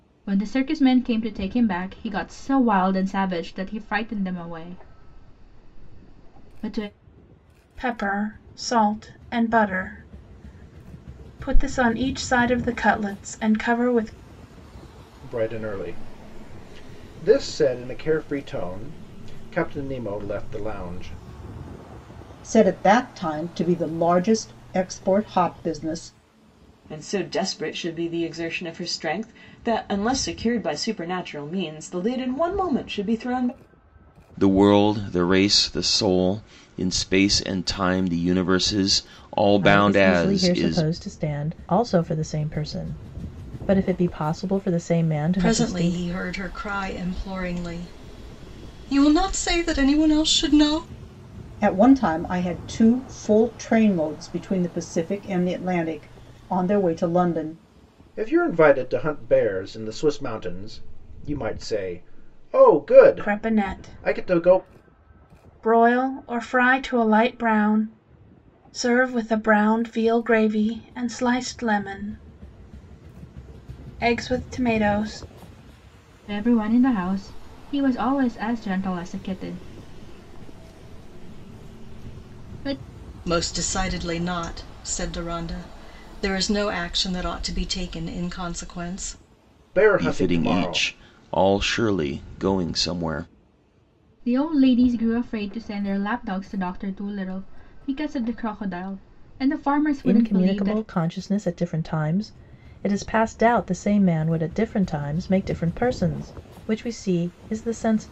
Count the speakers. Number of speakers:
8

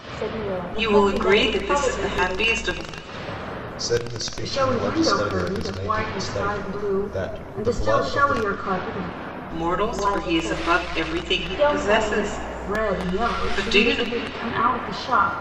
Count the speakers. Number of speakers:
4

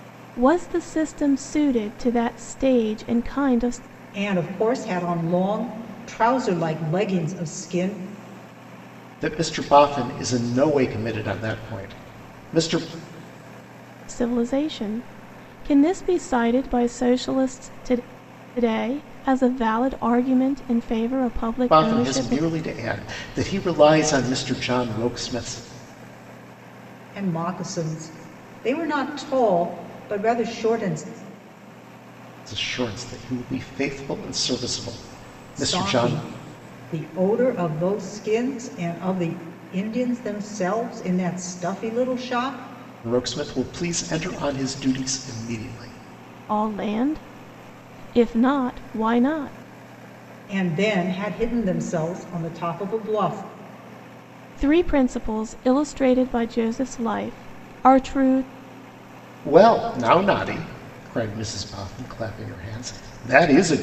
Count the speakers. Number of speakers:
3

